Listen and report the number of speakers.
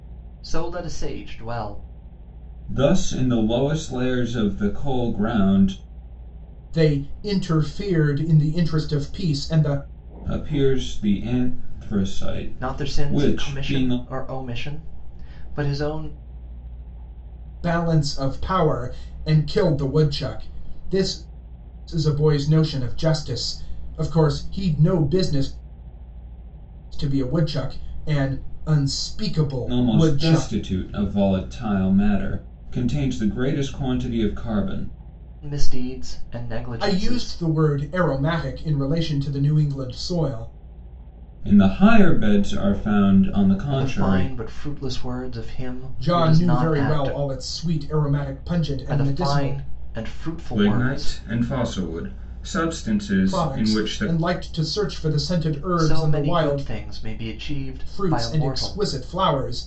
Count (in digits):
3